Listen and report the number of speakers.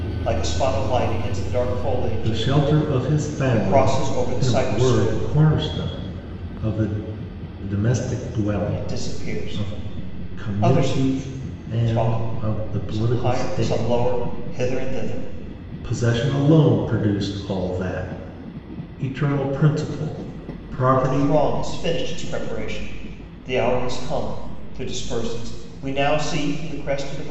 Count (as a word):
two